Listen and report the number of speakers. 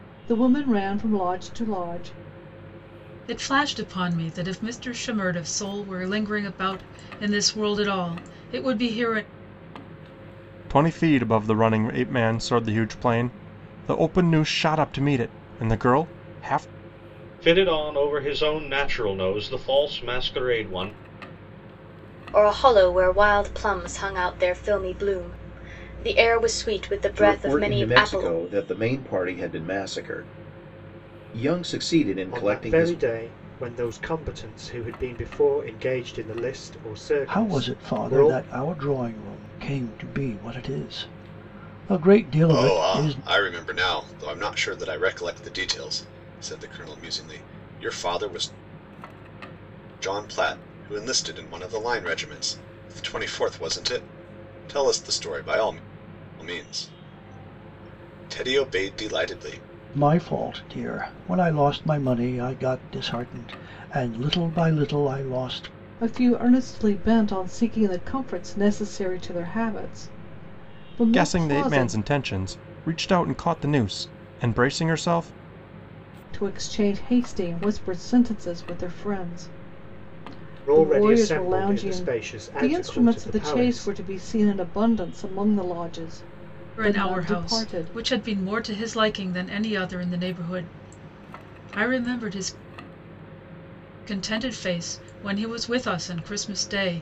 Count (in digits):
9